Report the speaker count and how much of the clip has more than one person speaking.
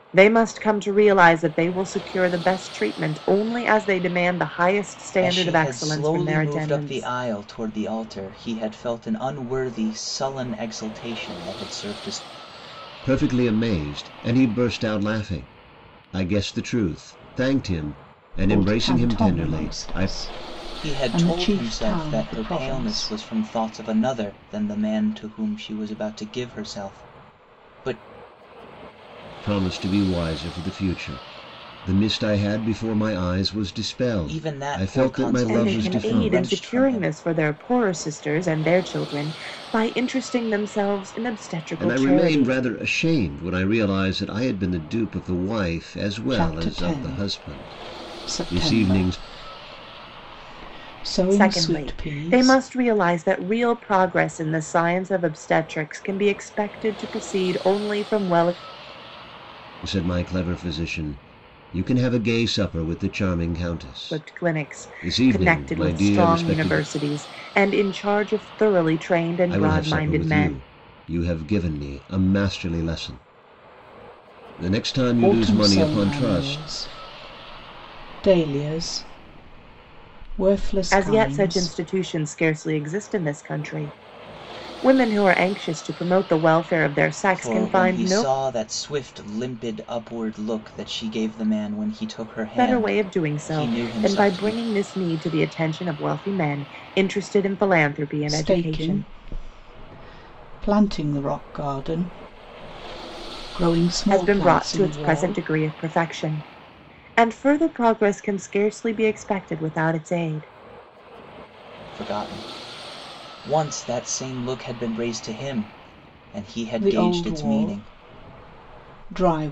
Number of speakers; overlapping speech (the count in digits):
4, about 23%